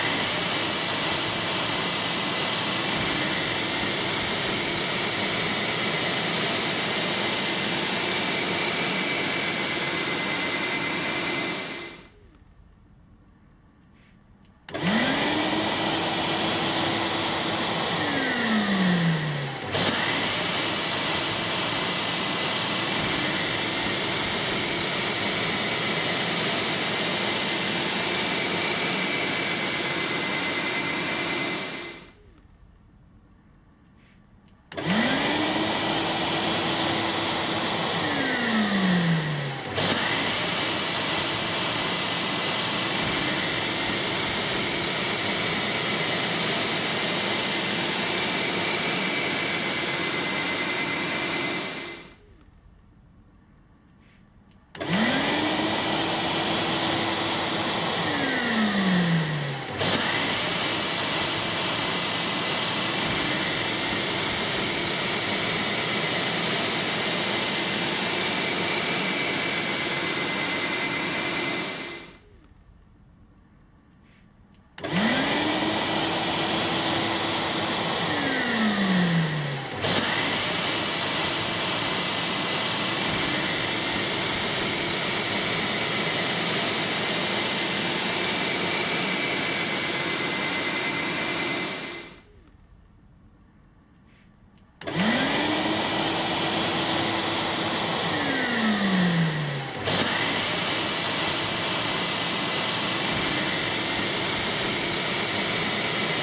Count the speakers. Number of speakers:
0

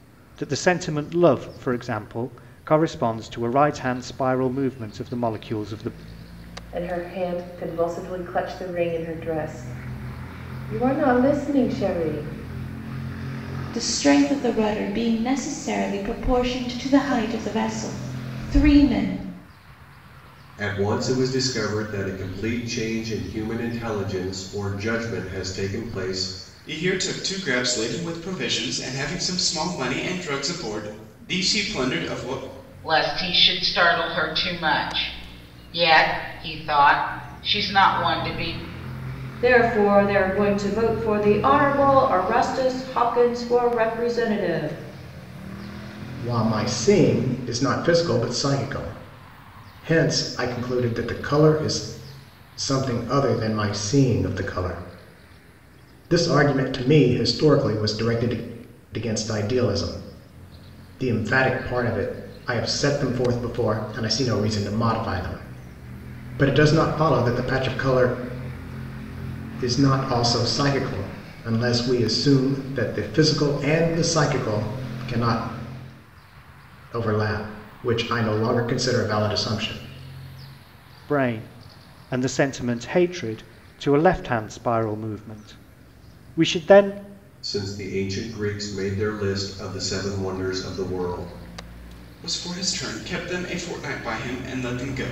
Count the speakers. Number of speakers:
8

